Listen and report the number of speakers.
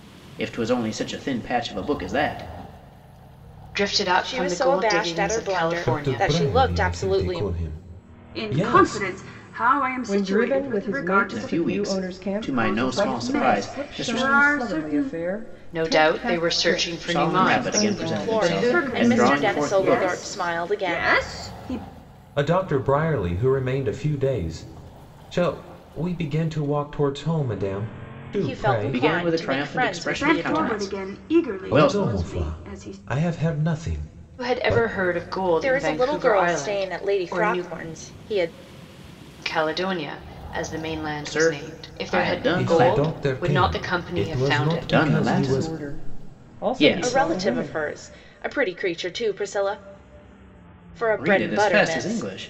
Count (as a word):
six